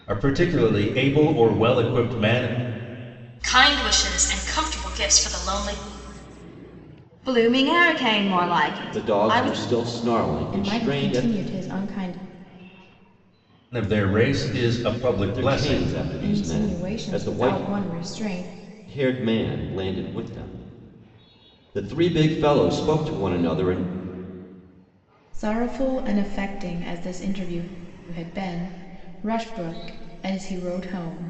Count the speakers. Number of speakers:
five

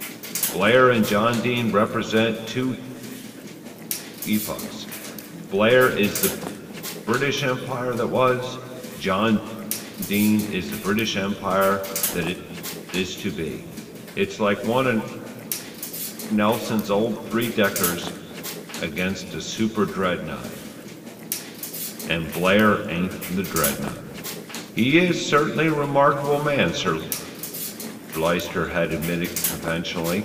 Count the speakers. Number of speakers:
one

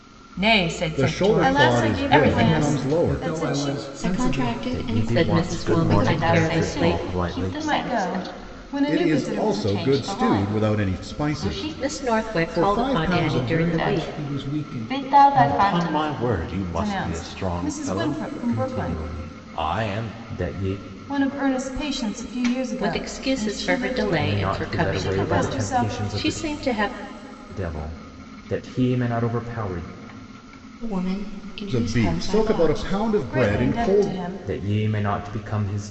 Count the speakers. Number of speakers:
nine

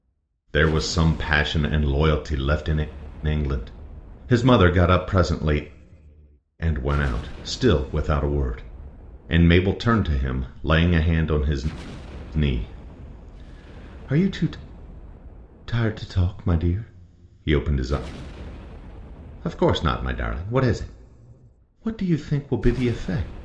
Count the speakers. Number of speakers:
one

